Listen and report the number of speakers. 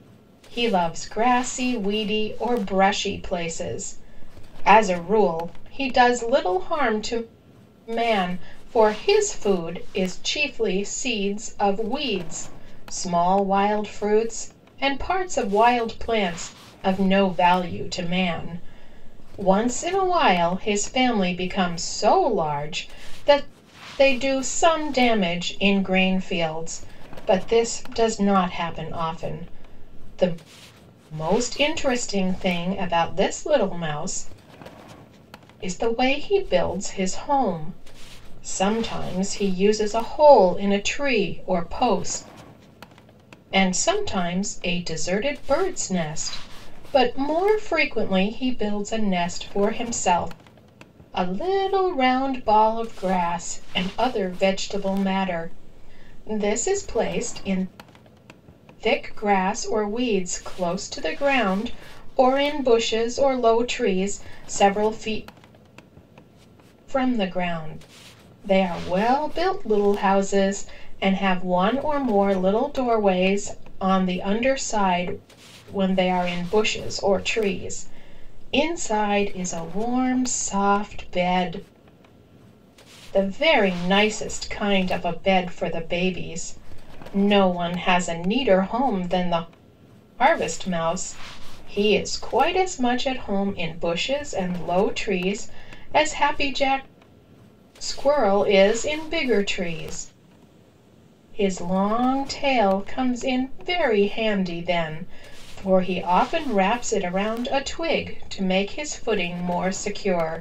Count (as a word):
one